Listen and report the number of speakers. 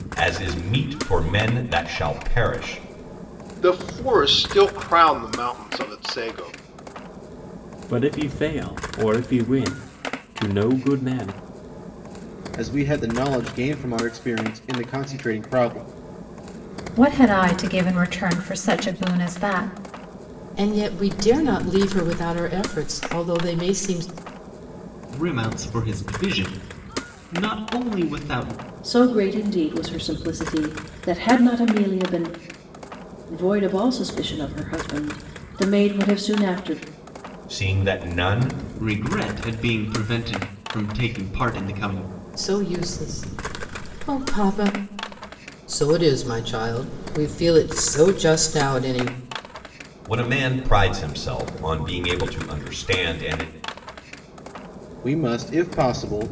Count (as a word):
eight